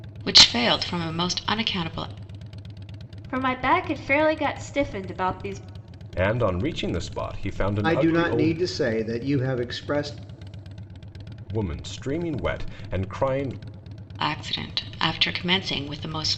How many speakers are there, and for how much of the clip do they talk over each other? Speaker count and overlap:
4, about 5%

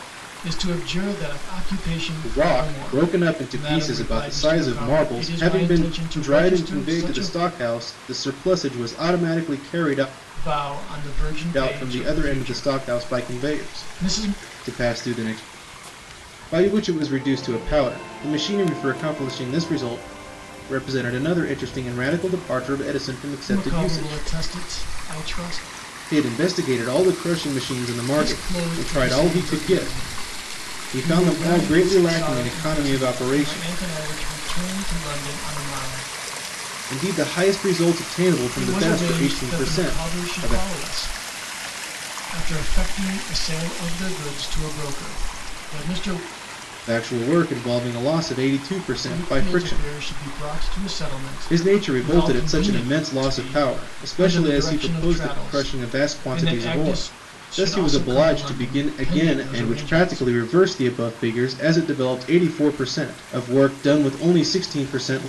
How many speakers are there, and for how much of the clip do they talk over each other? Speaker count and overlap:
2, about 36%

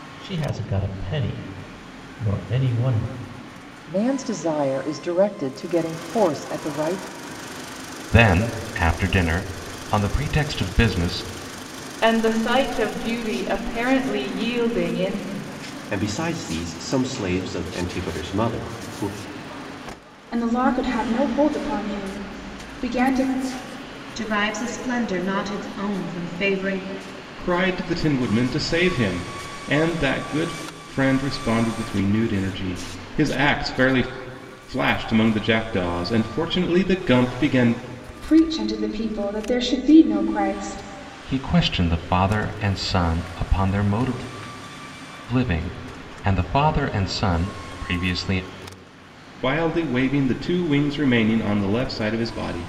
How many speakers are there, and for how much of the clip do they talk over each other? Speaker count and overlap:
8, no overlap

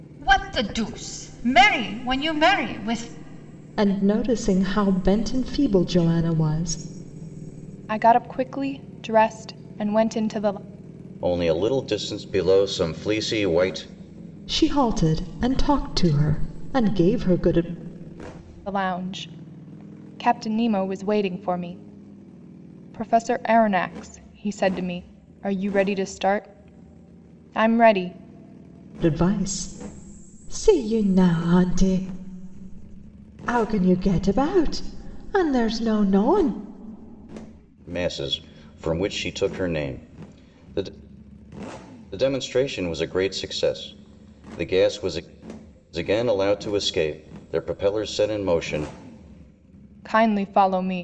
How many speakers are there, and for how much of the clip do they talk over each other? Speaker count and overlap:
4, no overlap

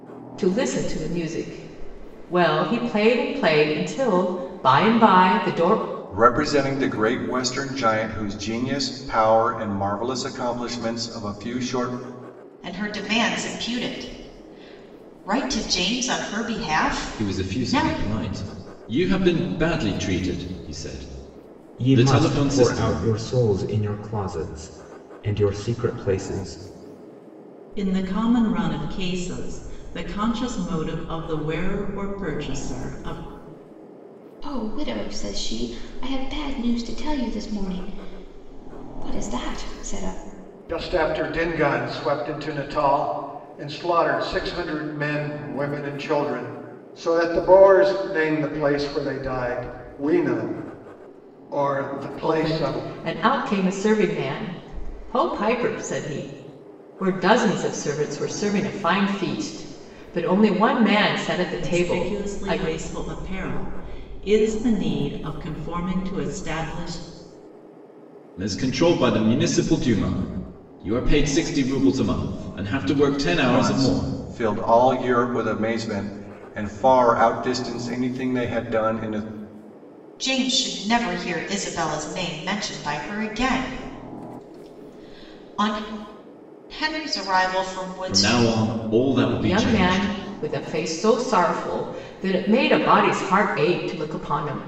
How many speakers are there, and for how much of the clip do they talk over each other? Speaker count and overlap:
8, about 6%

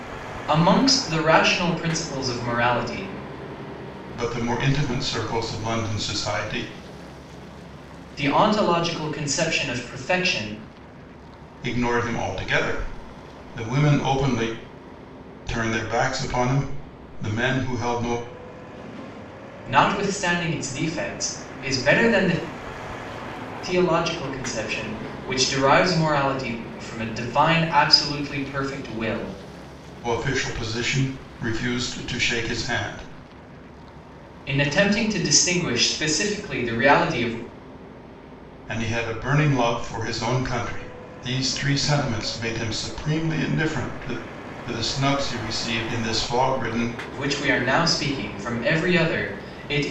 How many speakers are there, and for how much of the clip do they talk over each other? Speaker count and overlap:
2, no overlap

